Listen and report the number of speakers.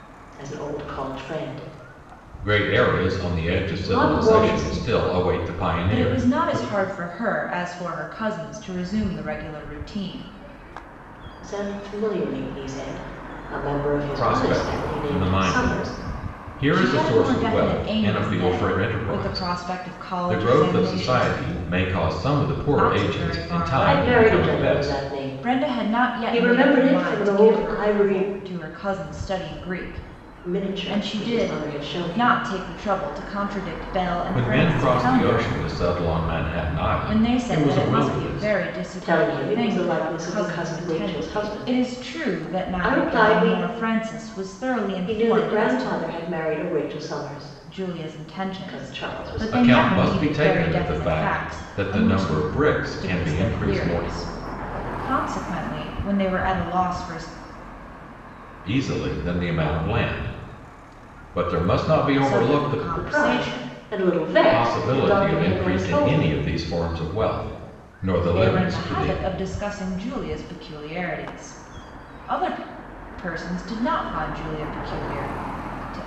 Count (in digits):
3